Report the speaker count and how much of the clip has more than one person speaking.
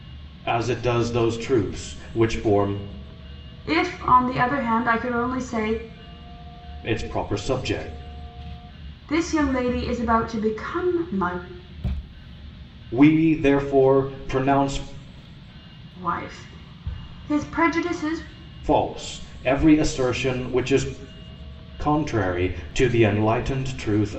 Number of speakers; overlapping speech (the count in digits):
2, no overlap